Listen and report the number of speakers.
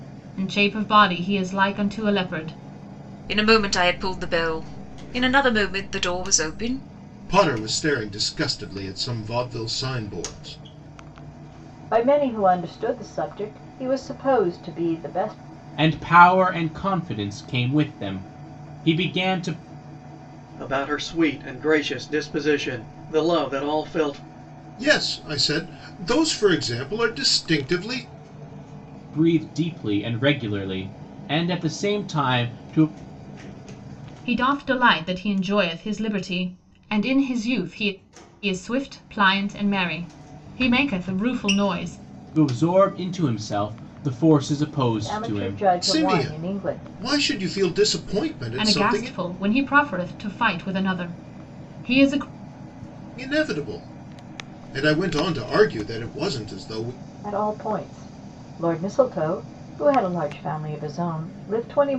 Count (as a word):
six